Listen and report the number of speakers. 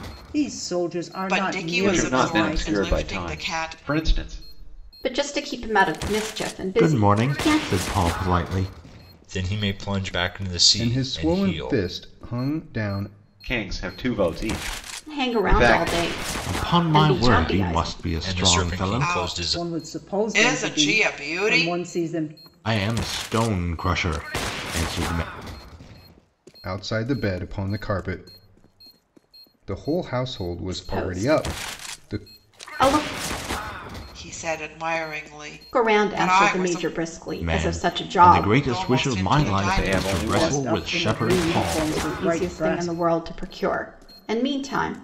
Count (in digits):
7